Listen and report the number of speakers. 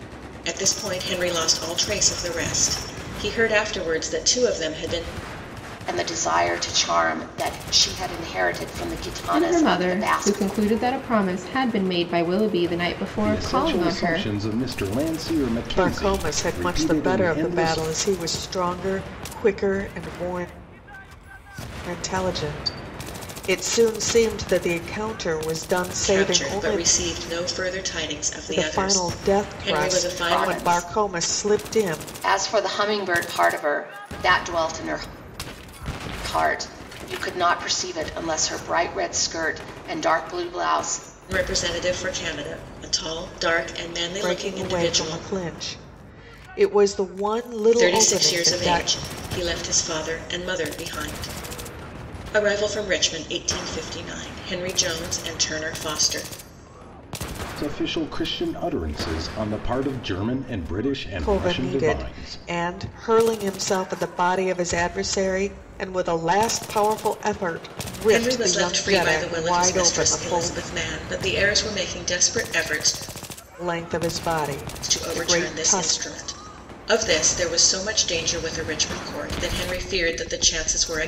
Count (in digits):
5